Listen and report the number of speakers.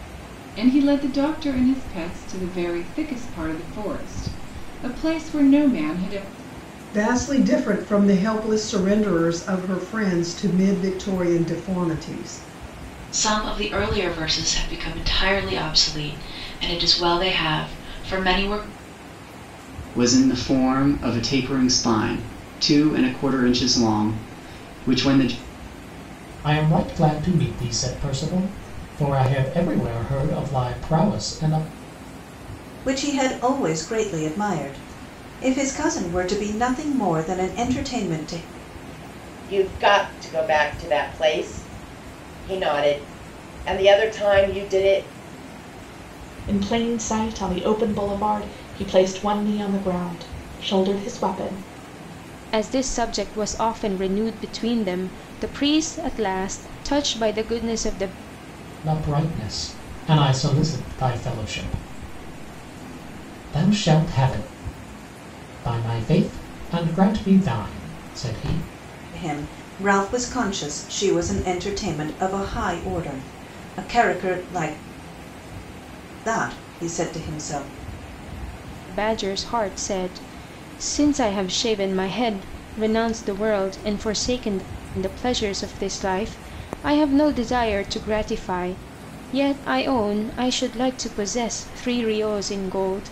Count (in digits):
9